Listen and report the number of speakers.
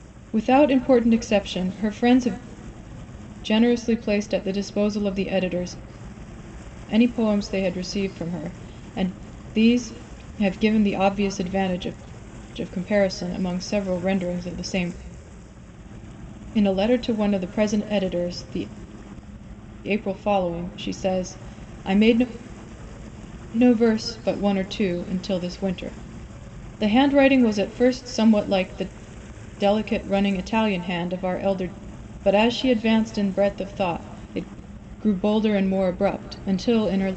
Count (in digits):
1